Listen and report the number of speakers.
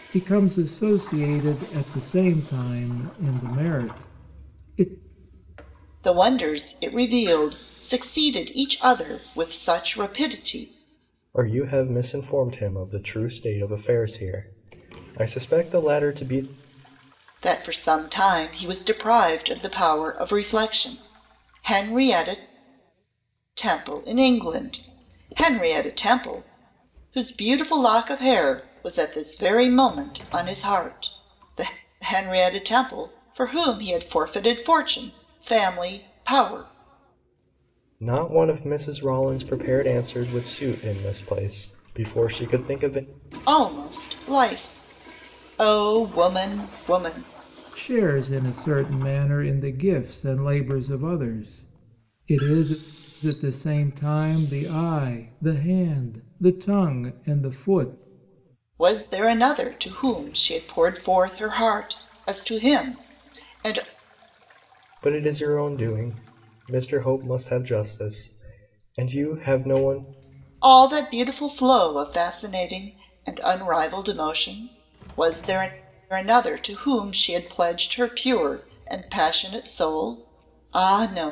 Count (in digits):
3